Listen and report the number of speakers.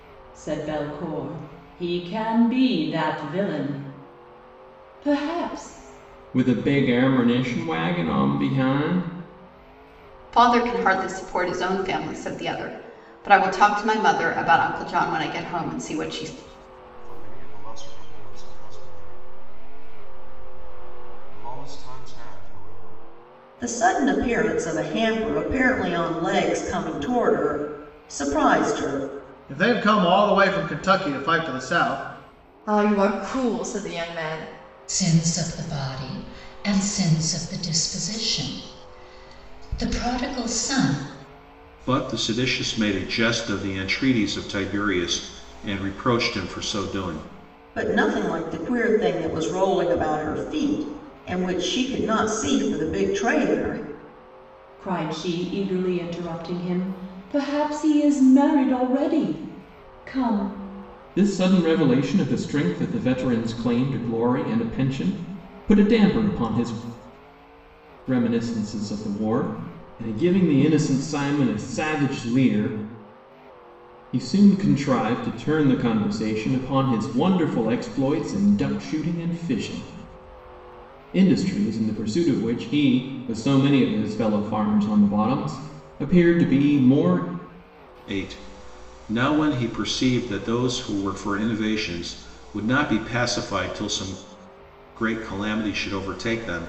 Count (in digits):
9